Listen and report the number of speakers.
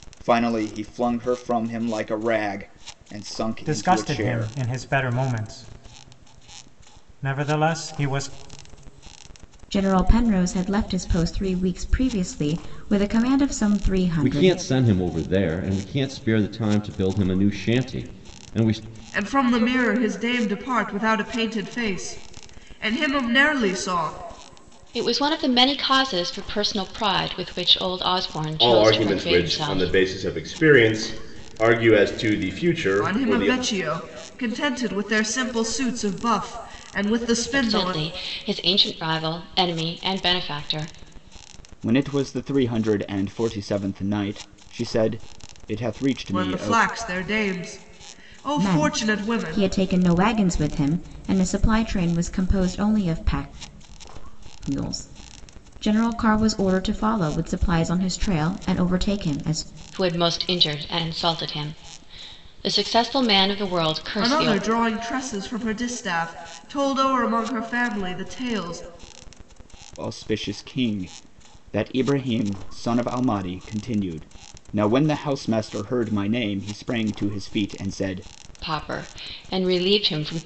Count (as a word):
seven